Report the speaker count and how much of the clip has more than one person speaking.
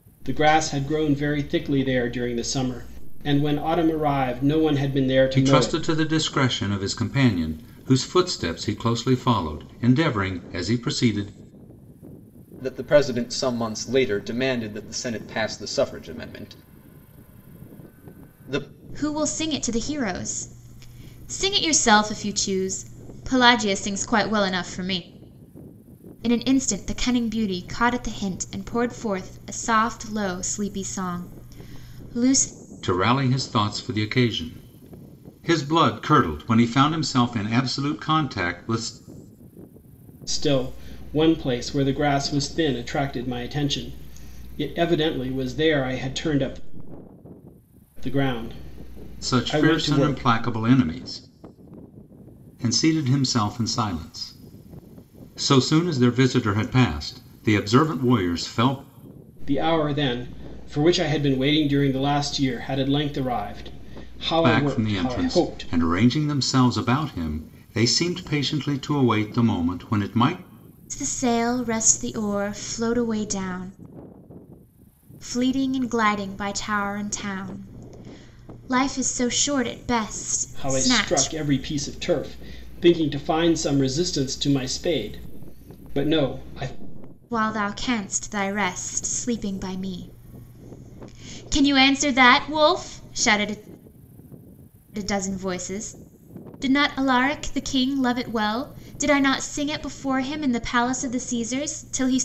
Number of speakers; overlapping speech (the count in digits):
4, about 4%